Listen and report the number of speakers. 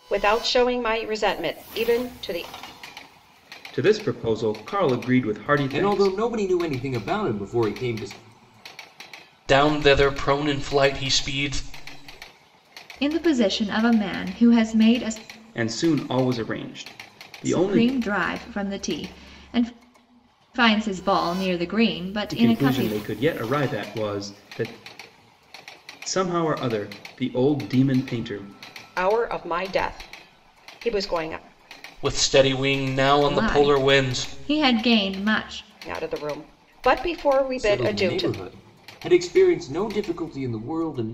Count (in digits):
5